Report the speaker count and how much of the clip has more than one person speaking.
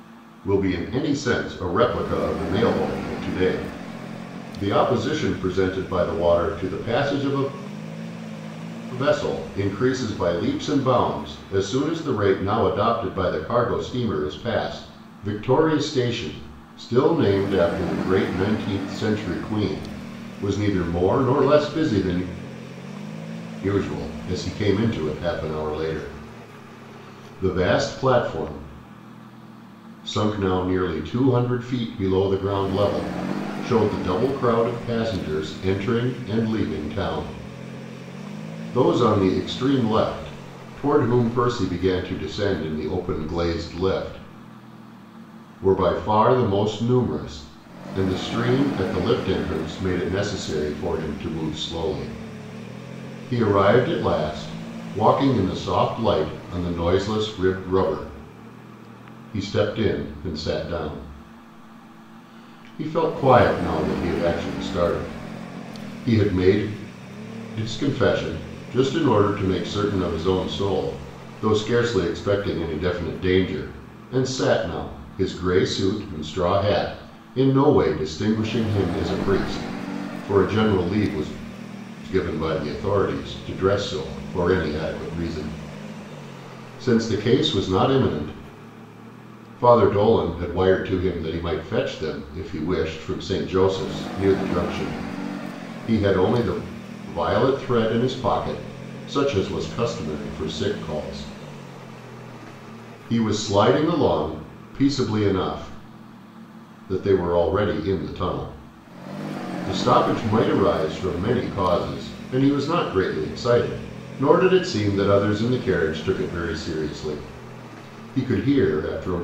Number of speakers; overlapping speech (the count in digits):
1, no overlap